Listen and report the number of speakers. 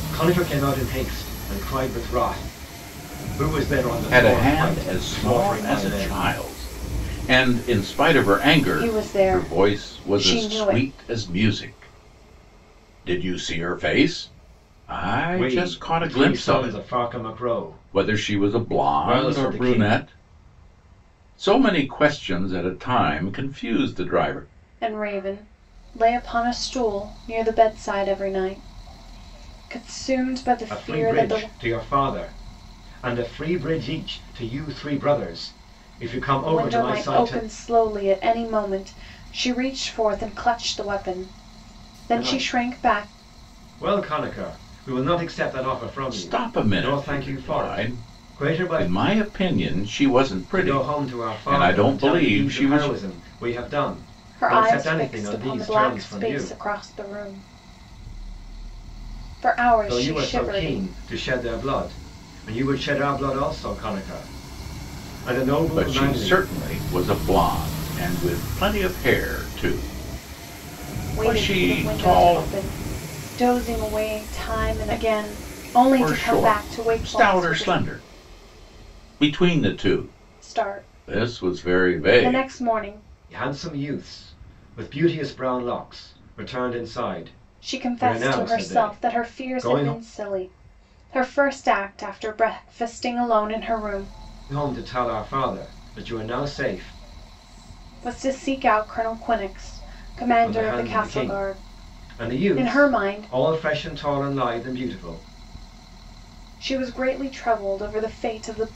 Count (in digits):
3